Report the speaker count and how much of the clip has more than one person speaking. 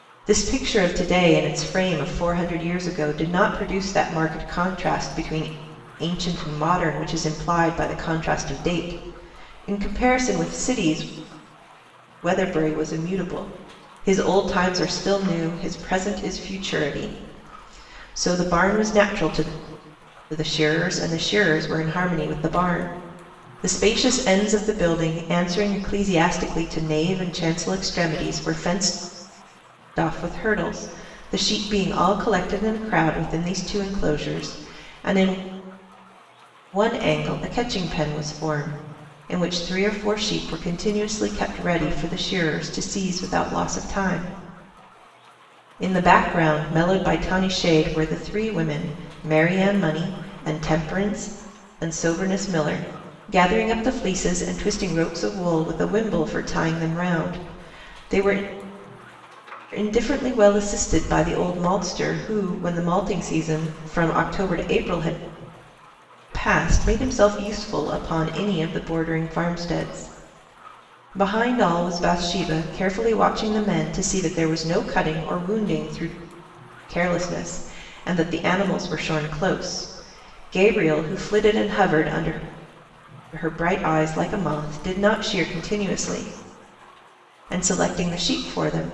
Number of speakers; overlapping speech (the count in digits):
1, no overlap